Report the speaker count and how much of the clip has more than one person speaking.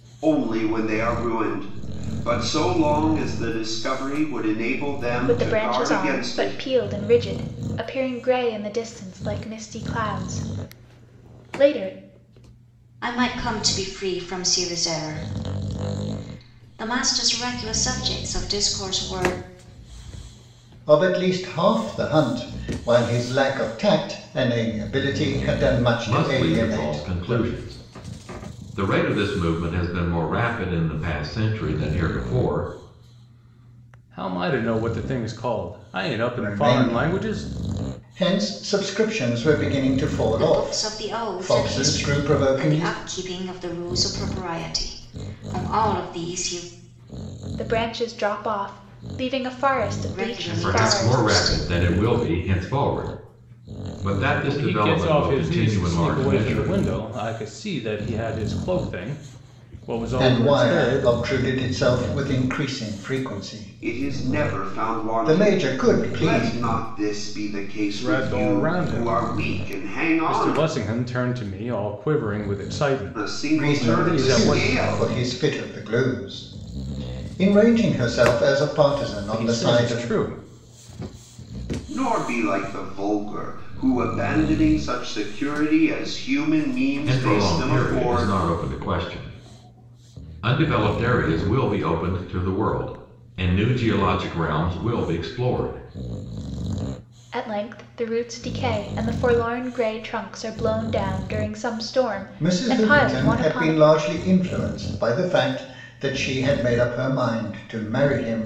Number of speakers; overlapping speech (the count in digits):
6, about 20%